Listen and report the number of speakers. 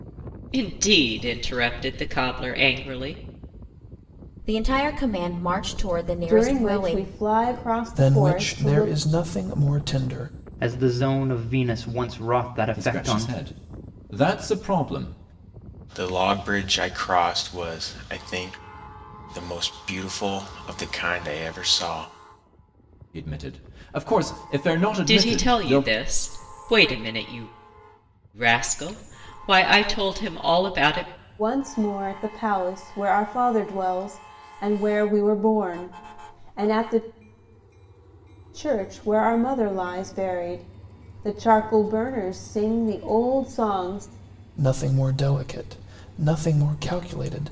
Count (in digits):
7